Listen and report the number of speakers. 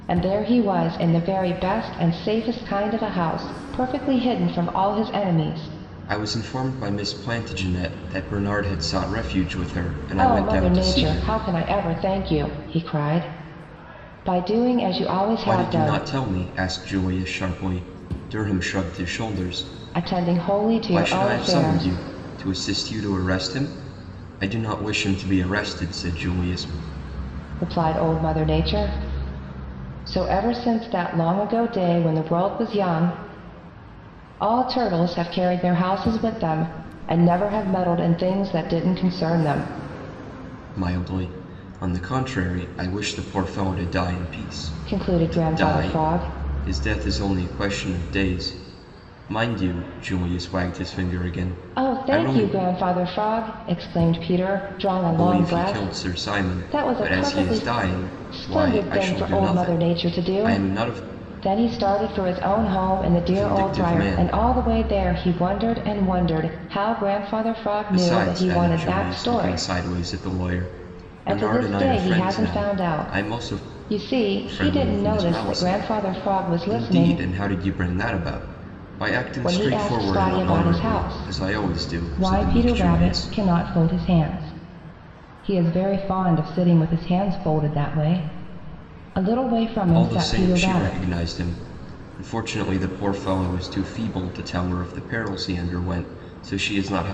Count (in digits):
2